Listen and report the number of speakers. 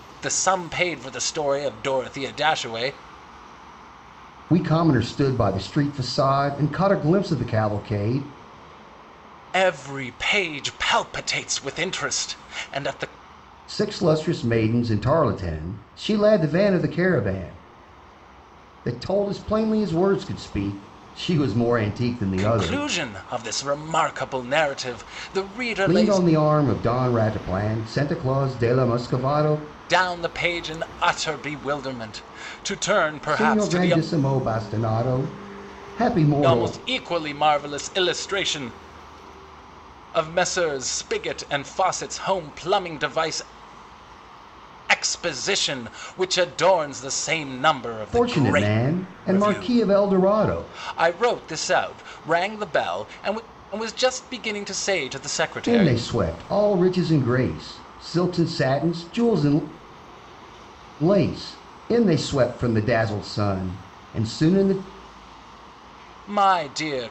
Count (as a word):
two